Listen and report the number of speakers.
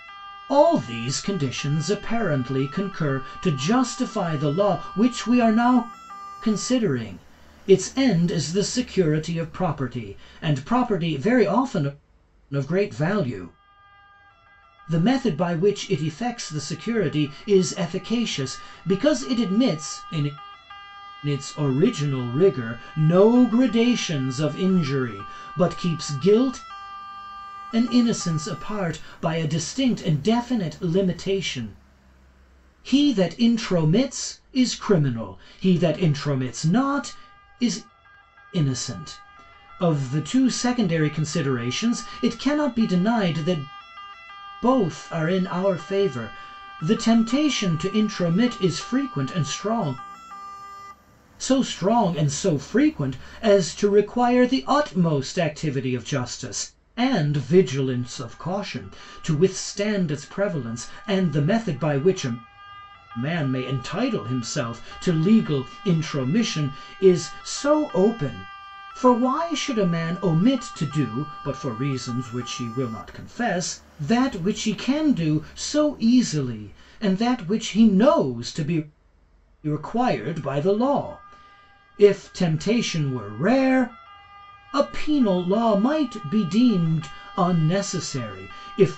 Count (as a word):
one